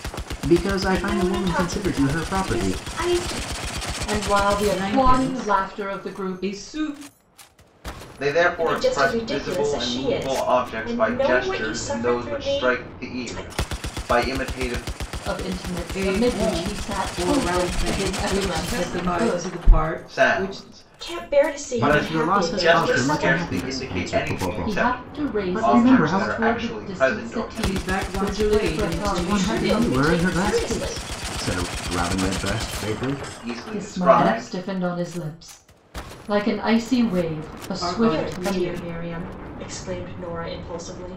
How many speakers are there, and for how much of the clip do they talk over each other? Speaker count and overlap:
5, about 61%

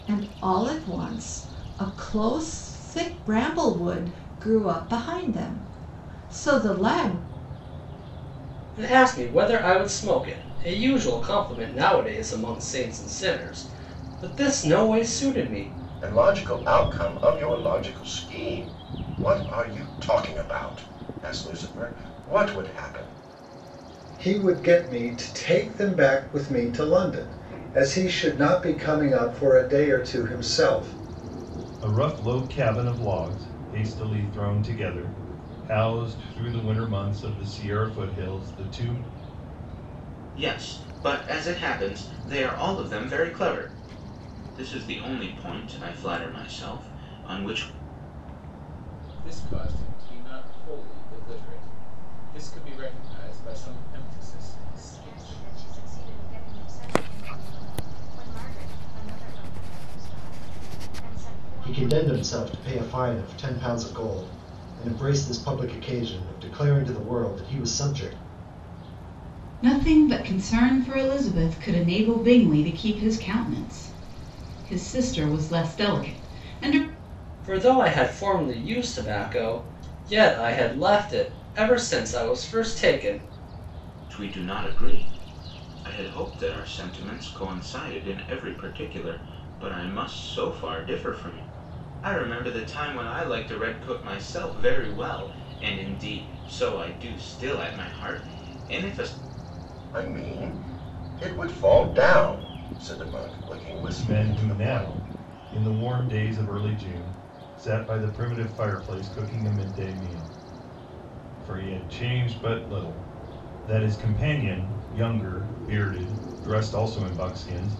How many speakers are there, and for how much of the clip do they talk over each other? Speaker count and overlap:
10, about 2%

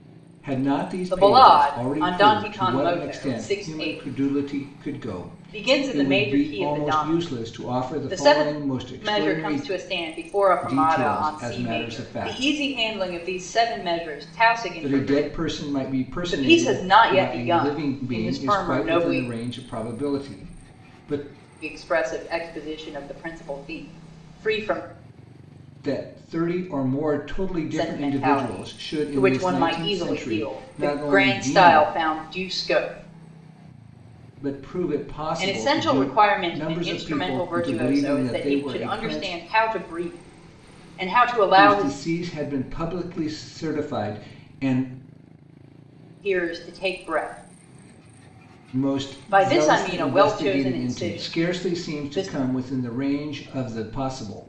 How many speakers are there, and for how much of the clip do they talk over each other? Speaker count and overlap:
2, about 45%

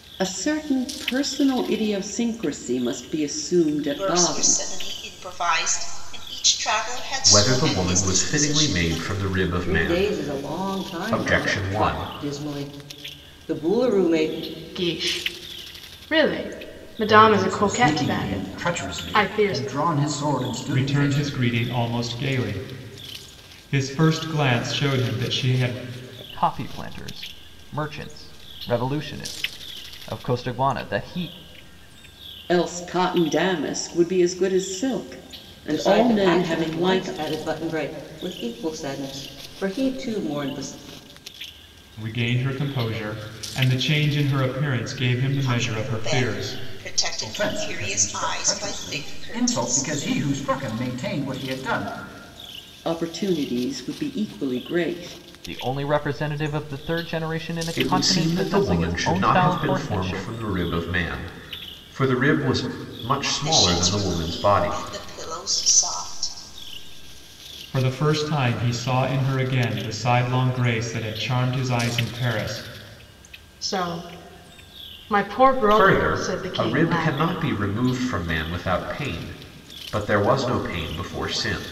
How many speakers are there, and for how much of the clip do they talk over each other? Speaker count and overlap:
8, about 24%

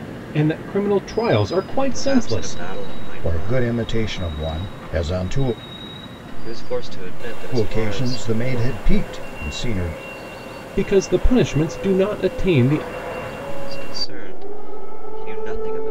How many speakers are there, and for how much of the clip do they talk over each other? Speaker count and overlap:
3, about 16%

